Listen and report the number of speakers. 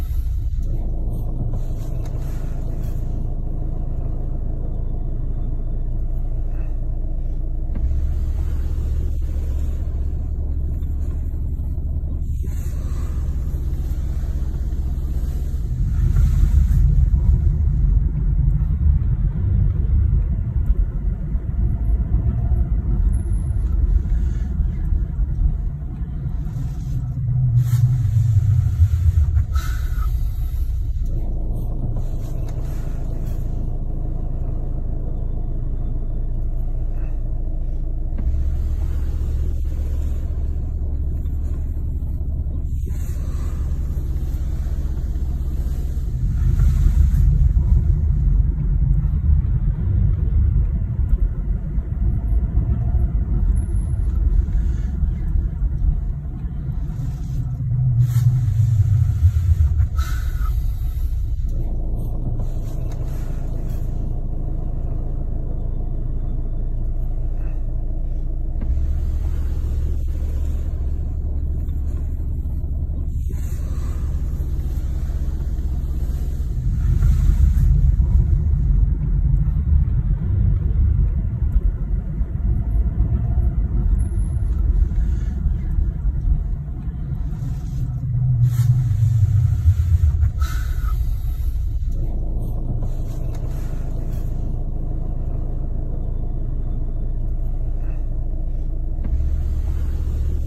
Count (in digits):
0